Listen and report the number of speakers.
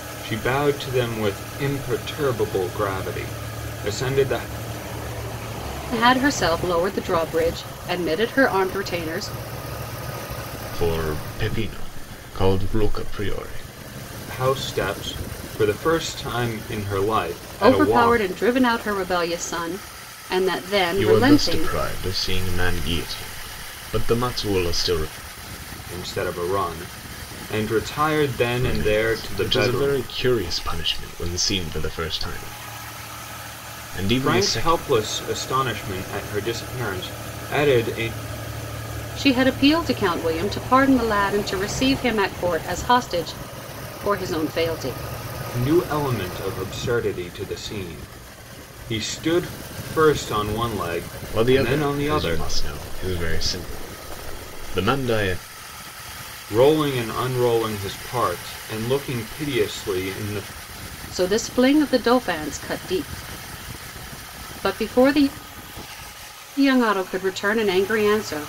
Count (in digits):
3